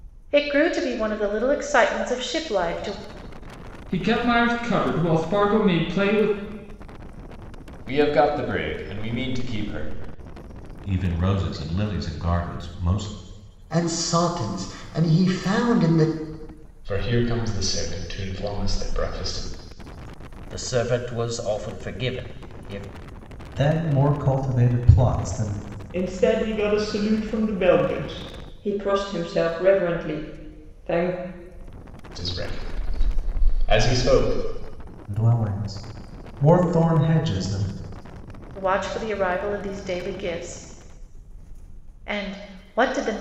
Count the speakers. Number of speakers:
9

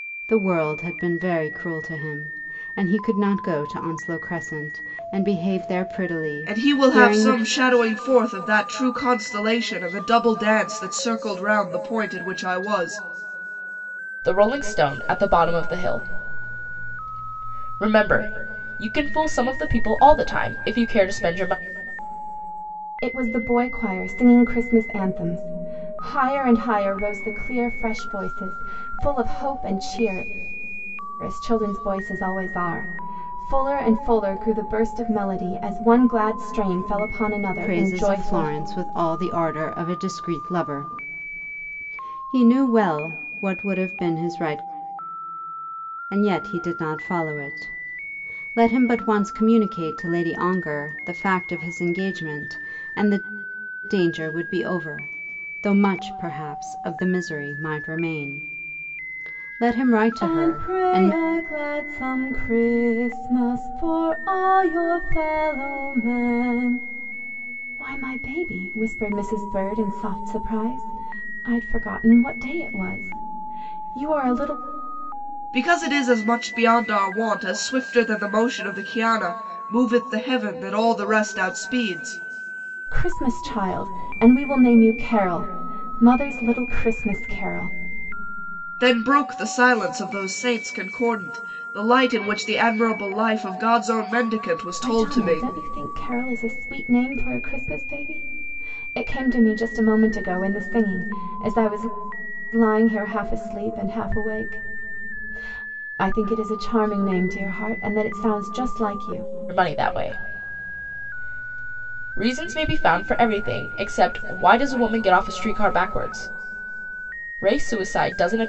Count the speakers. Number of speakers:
4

